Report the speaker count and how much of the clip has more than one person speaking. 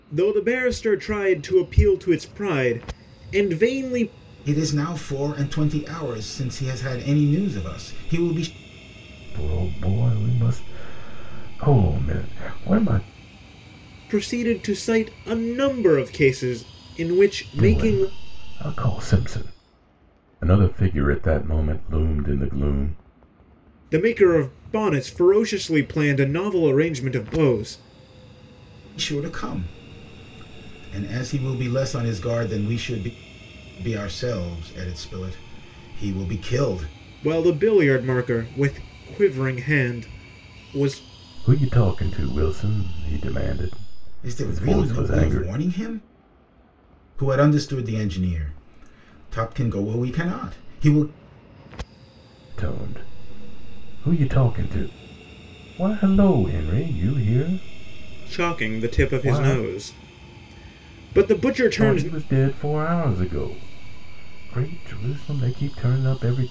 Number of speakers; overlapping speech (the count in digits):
3, about 6%